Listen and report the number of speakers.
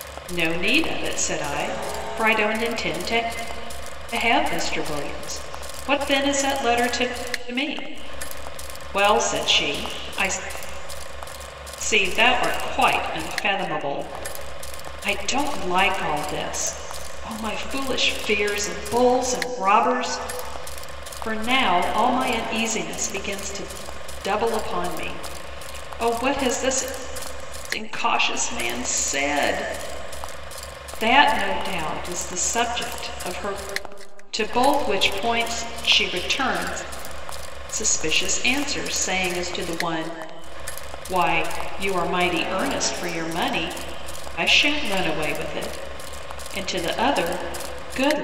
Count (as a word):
one